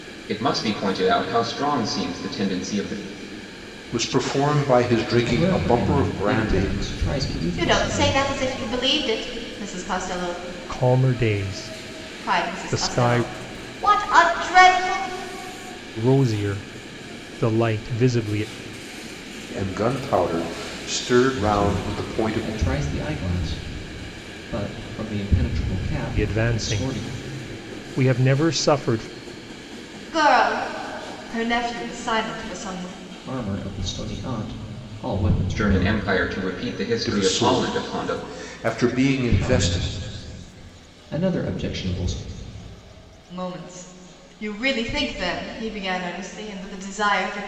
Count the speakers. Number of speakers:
5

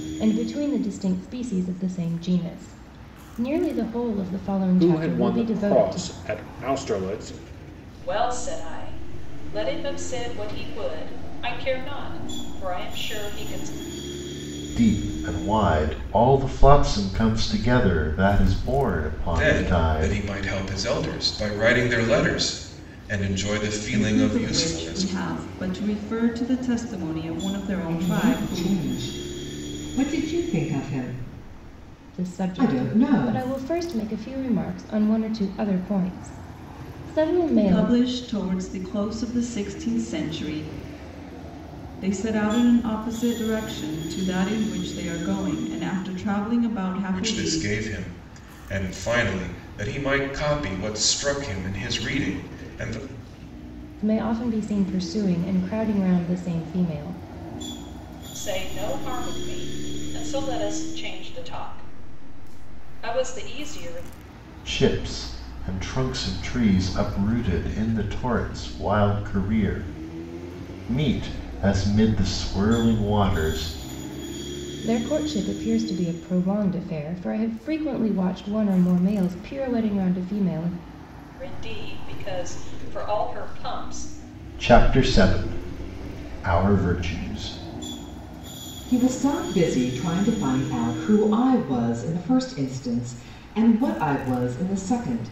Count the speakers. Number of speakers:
7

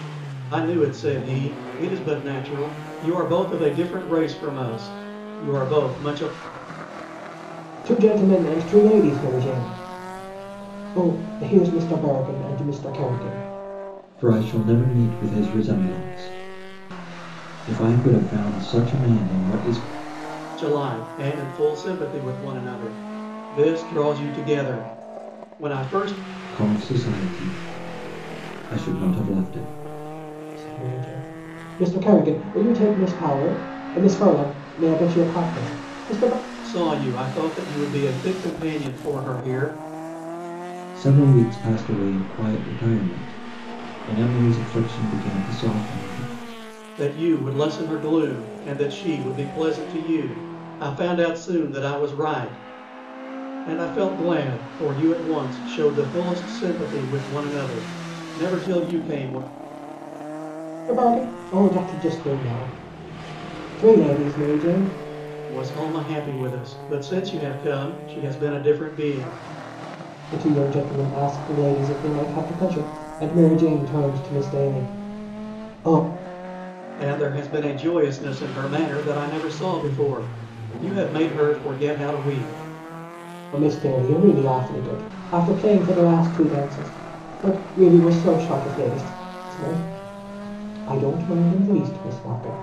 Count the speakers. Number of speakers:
3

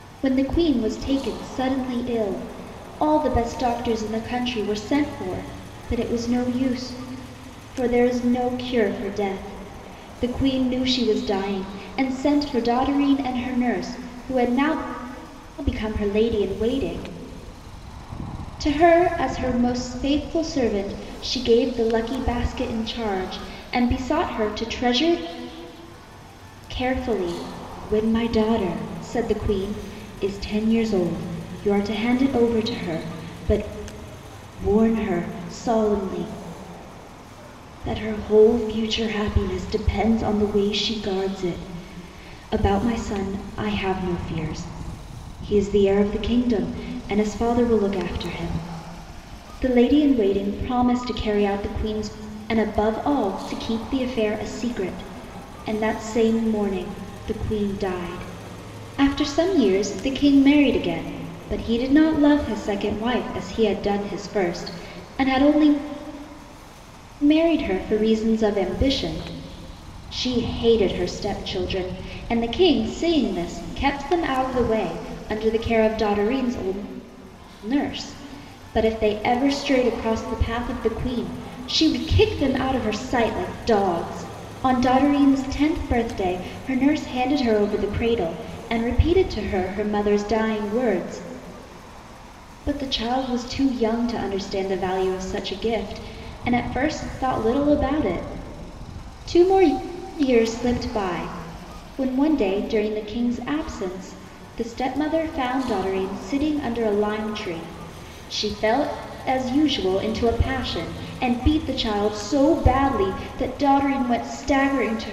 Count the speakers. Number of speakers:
1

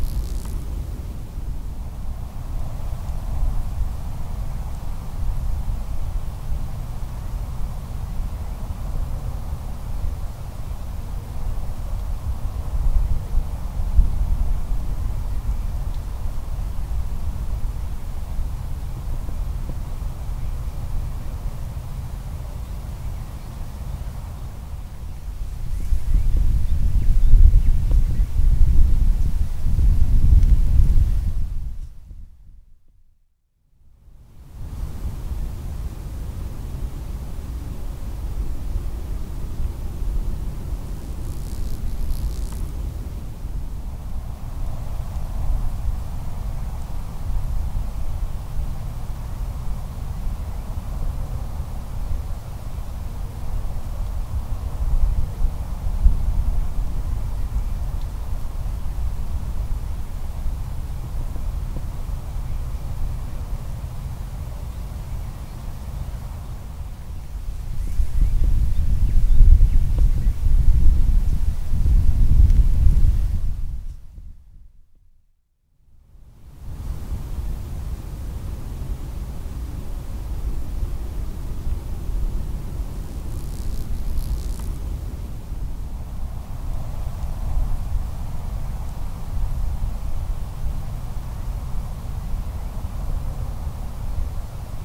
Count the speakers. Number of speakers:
0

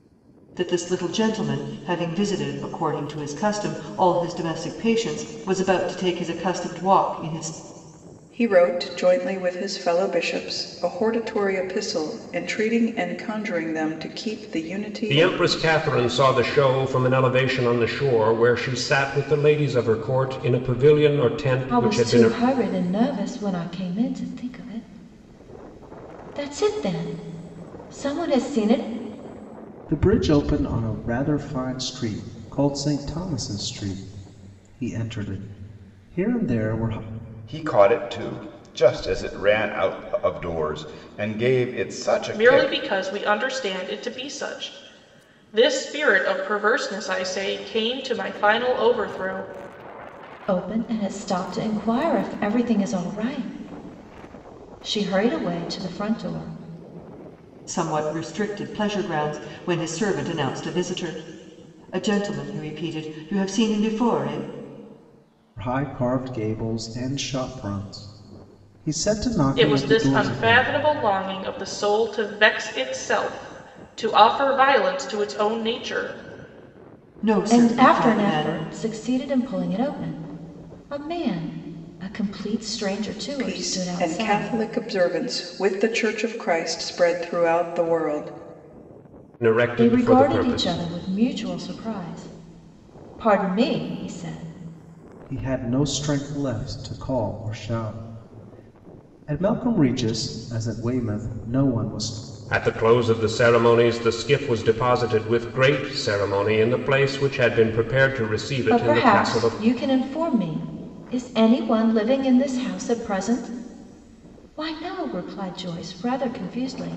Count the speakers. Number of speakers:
7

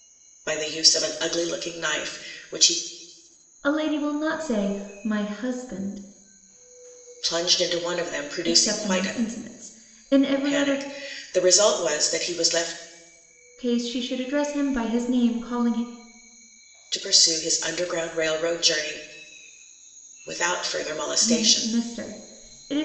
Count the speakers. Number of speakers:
2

